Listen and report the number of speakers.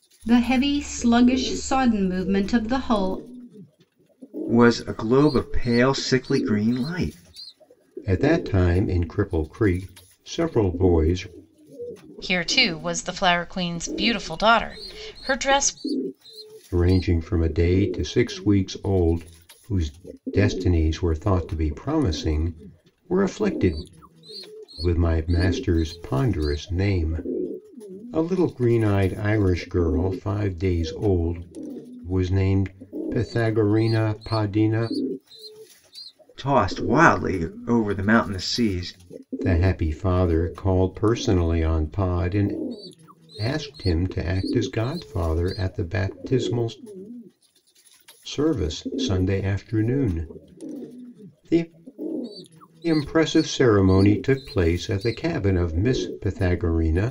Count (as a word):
four